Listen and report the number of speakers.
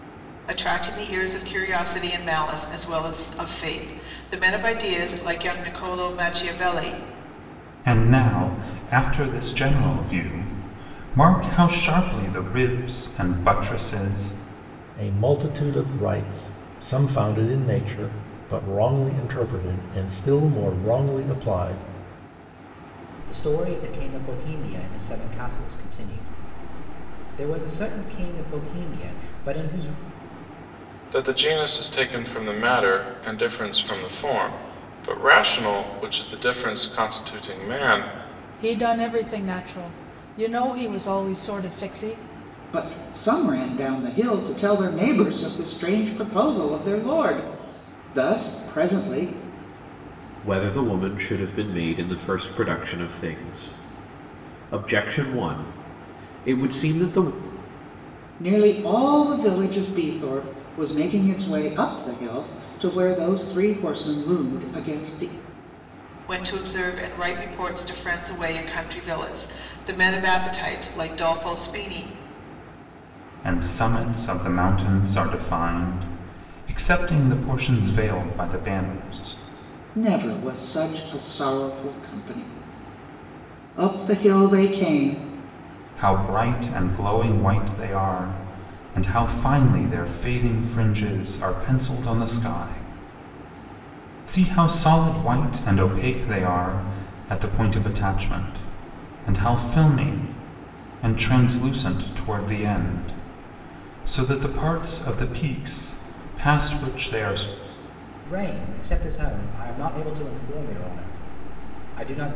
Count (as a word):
eight